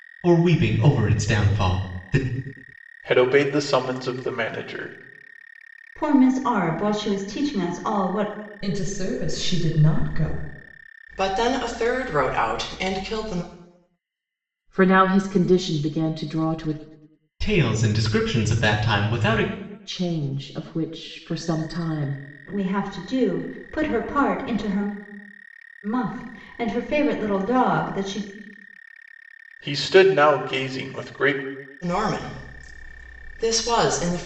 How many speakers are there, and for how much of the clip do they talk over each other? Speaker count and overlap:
six, no overlap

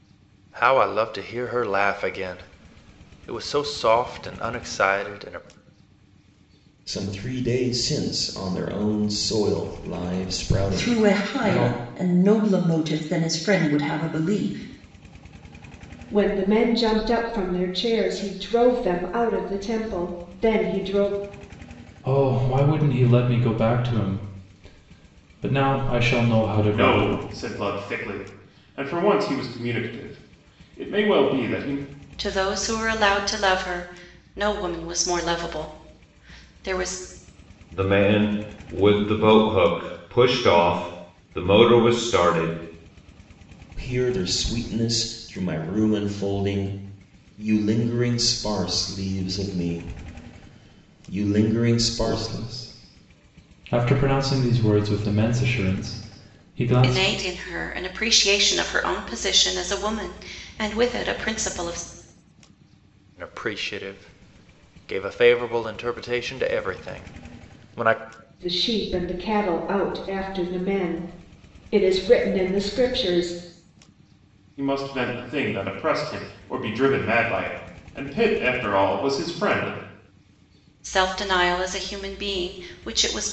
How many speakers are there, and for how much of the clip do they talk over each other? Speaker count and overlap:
eight, about 3%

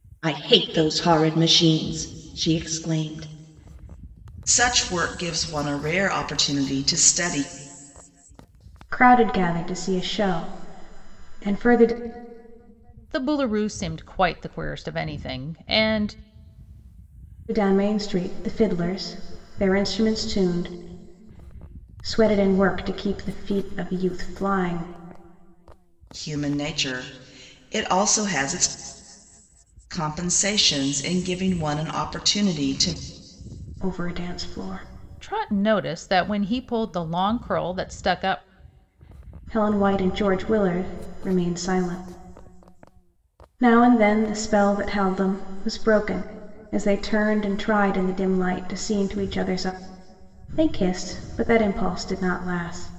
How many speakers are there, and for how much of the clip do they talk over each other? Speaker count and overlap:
four, no overlap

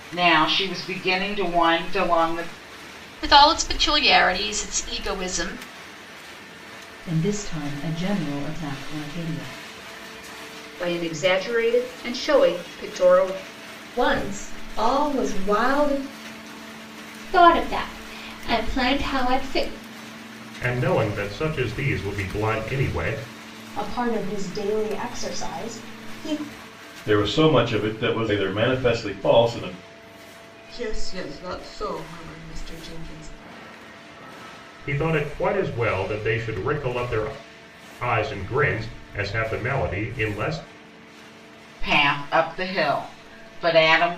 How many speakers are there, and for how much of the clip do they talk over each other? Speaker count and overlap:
ten, no overlap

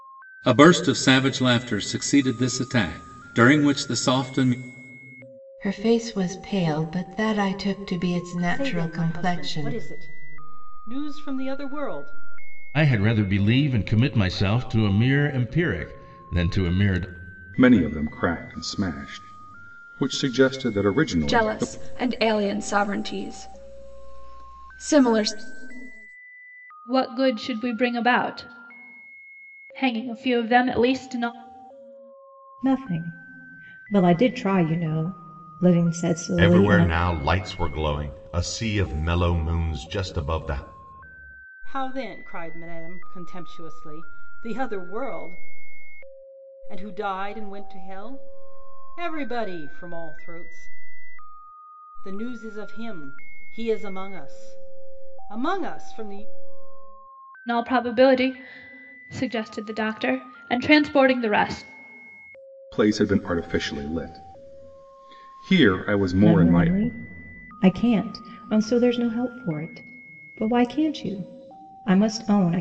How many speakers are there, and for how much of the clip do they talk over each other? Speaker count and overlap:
nine, about 4%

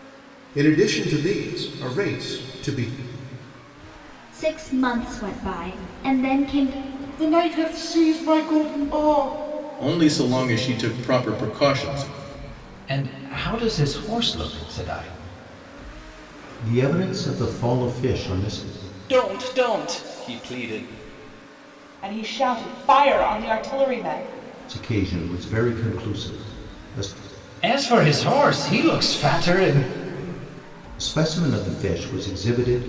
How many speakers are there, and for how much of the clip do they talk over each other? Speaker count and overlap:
eight, no overlap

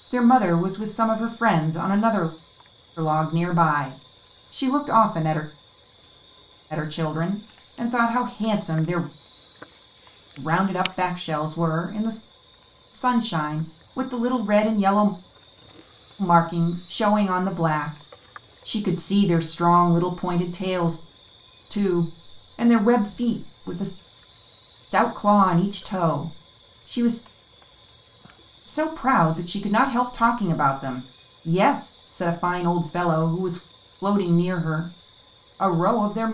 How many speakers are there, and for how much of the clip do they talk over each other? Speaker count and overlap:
one, no overlap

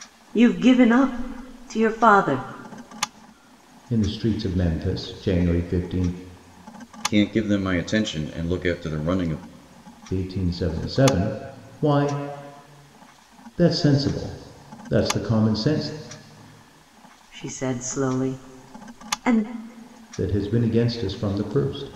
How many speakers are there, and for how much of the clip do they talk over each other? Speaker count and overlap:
three, no overlap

